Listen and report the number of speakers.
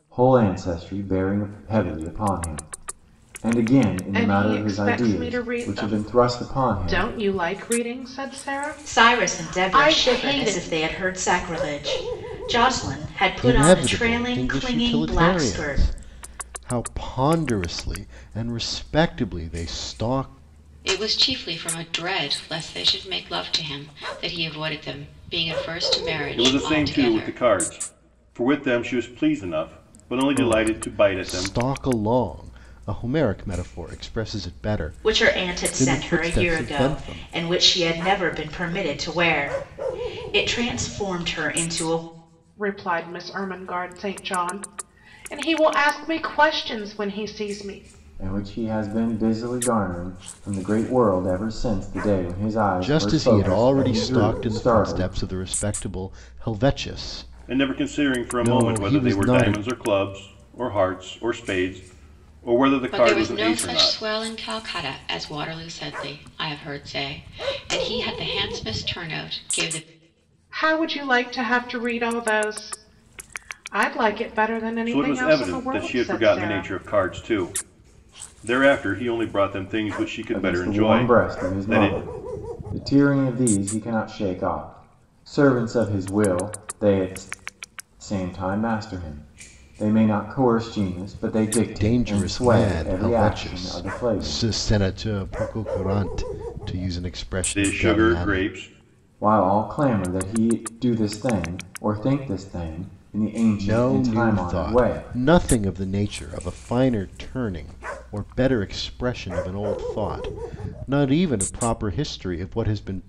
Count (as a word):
six